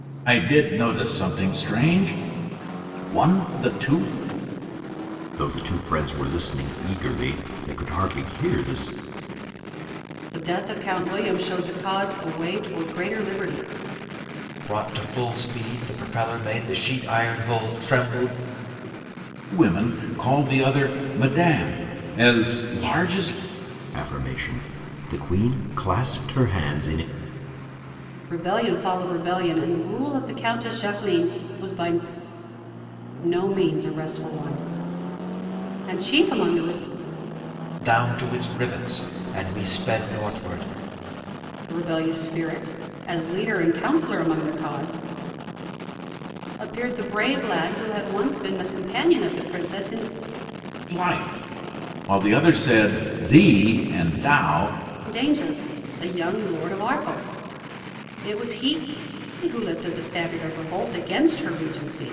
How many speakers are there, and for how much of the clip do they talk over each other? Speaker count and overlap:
4, no overlap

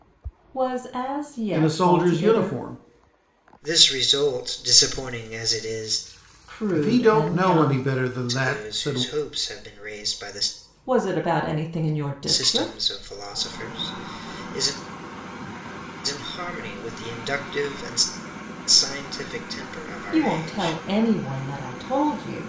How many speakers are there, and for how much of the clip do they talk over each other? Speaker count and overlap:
3, about 20%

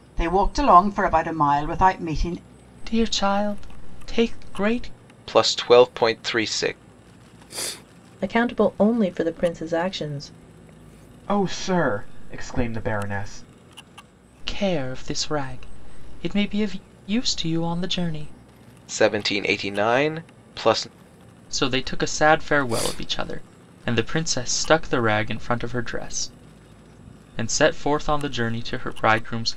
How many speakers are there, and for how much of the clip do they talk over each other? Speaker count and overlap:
5, no overlap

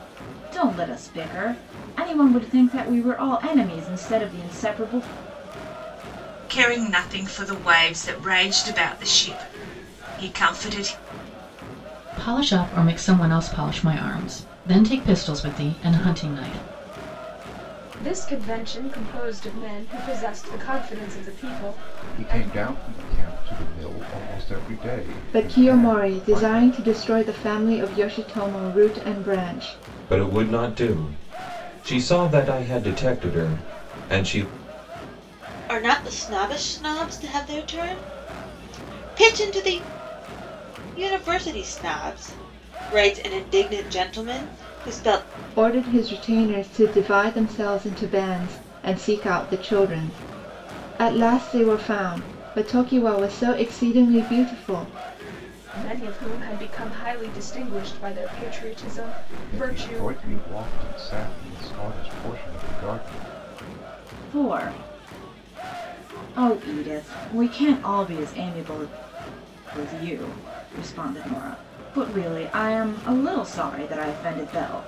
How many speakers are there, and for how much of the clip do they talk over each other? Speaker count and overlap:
8, about 4%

